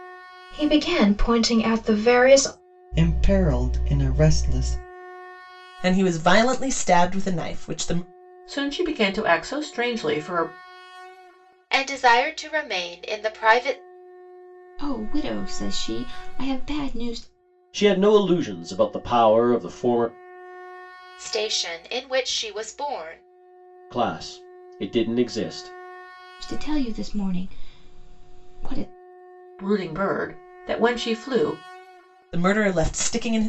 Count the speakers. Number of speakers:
7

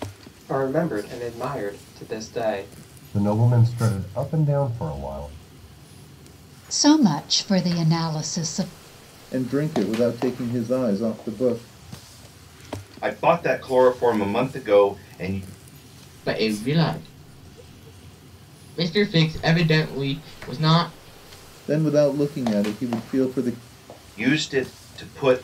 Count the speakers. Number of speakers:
6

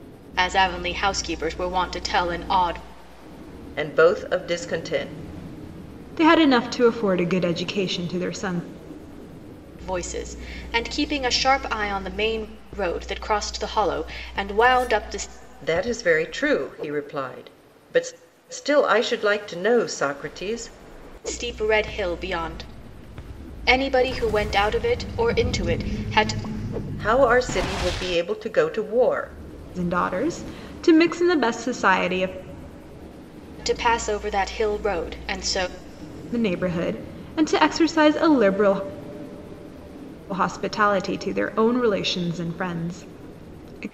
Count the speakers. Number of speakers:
3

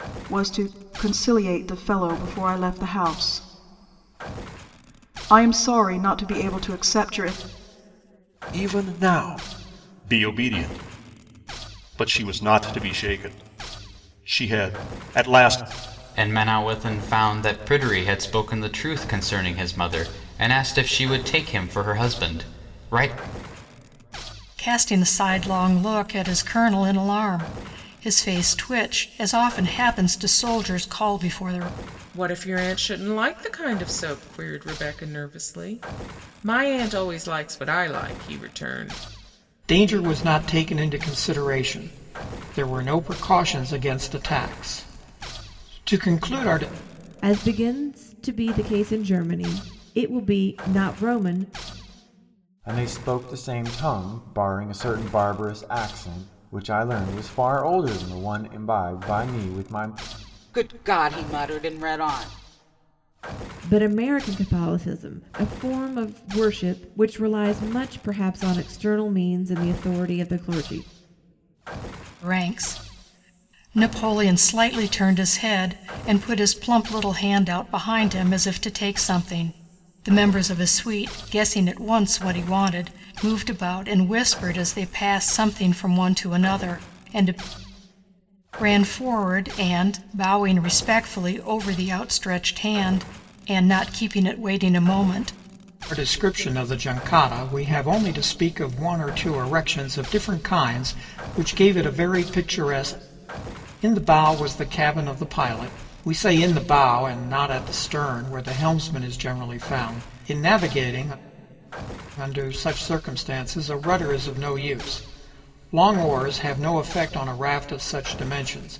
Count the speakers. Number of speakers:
9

